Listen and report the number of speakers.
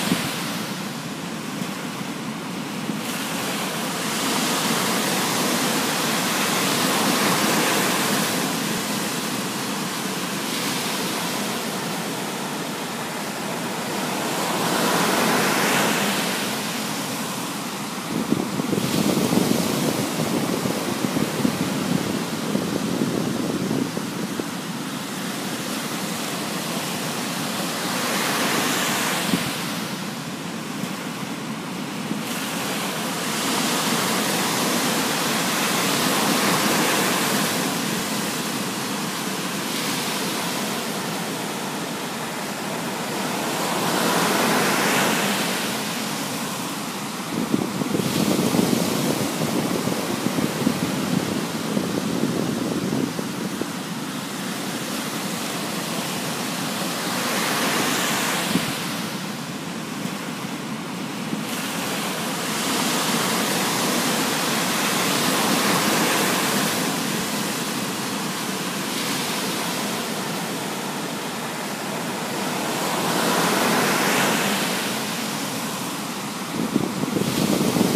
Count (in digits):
0